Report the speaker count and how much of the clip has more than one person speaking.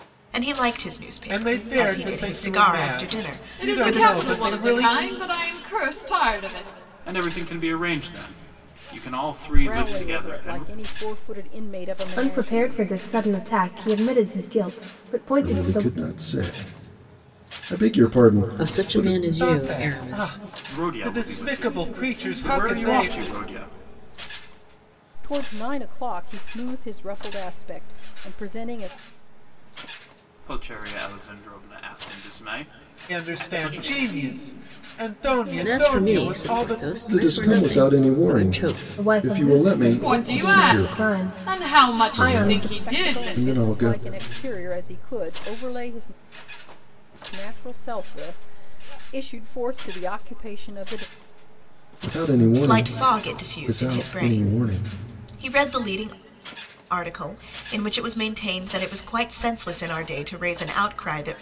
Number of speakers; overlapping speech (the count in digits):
8, about 35%